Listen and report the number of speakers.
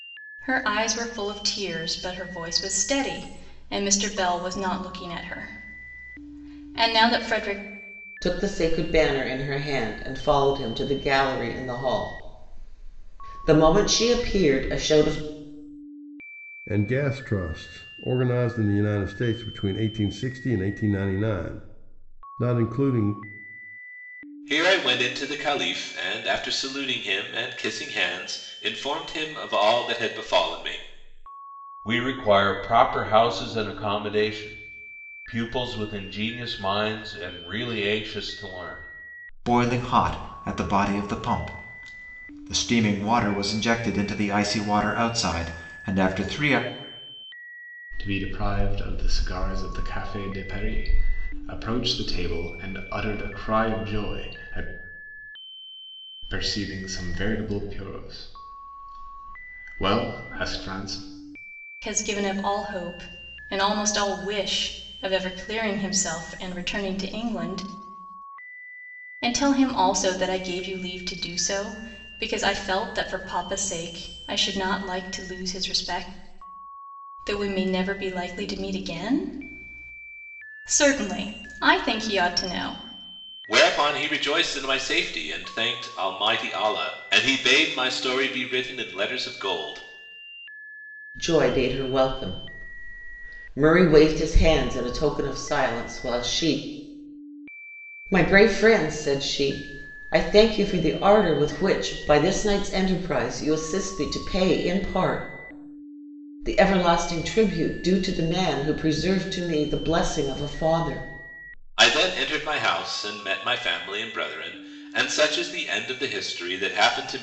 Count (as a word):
seven